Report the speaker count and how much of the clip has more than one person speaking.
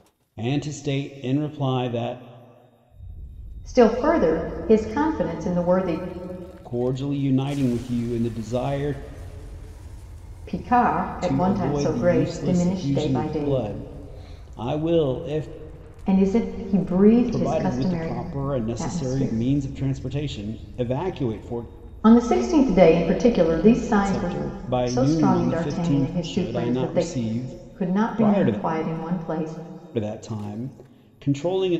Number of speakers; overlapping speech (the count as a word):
two, about 24%